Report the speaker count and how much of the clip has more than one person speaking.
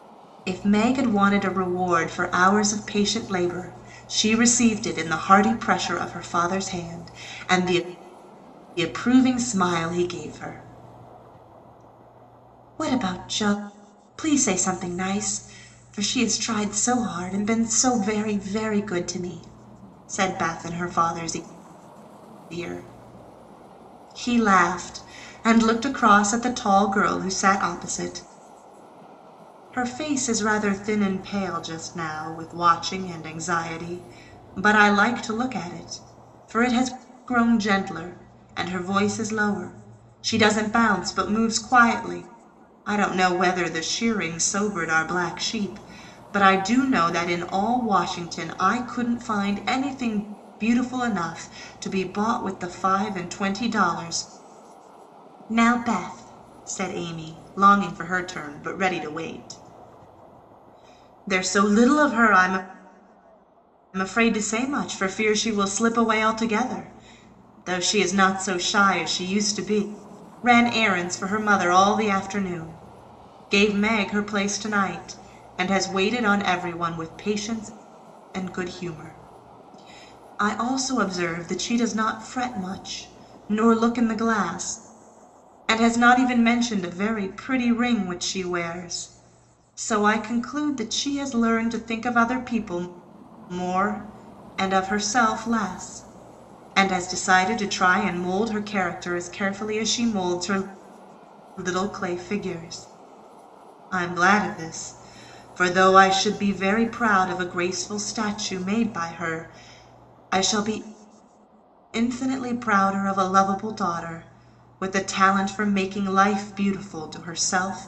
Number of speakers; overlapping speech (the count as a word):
one, no overlap